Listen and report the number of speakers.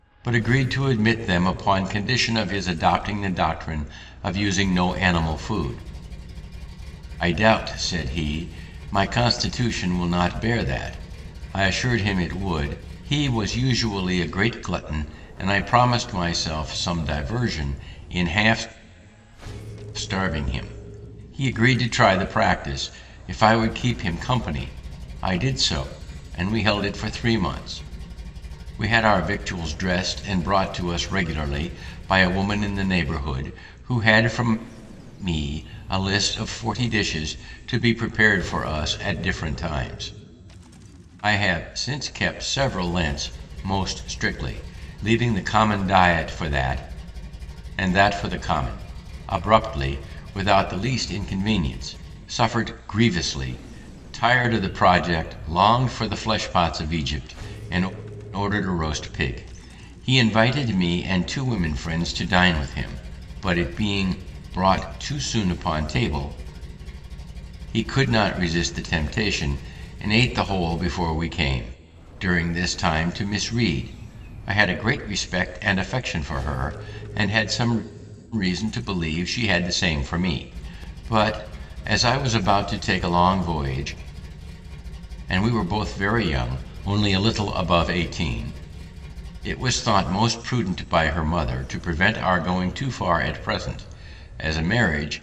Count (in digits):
1